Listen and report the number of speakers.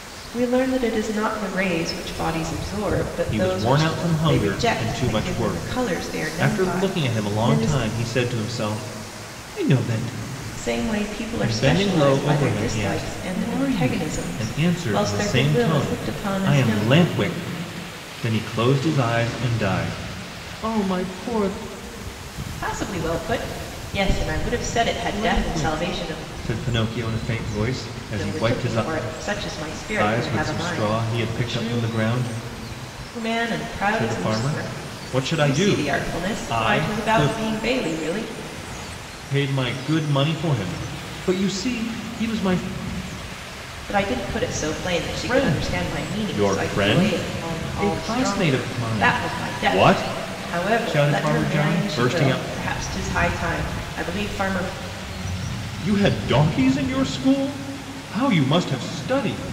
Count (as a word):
two